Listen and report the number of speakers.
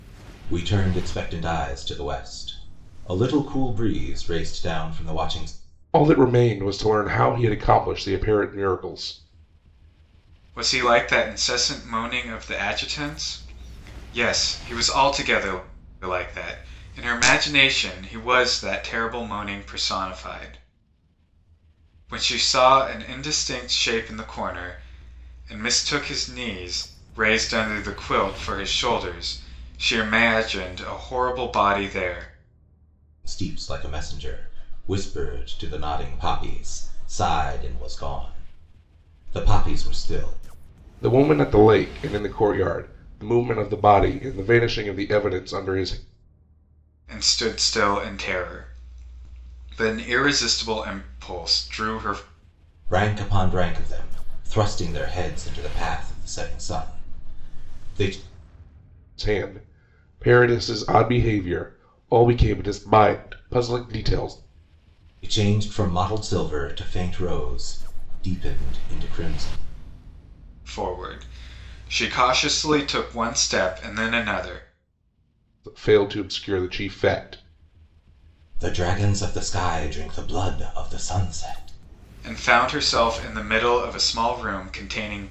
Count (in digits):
3